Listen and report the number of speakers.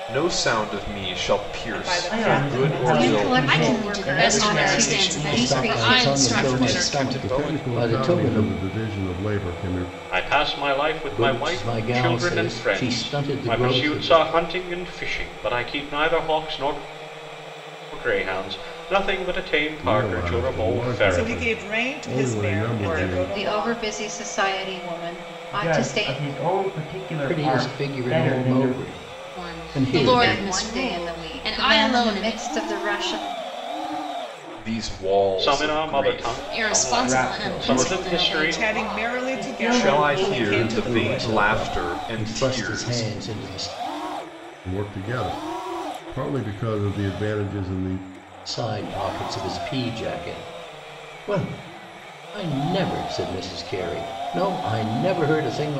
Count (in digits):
9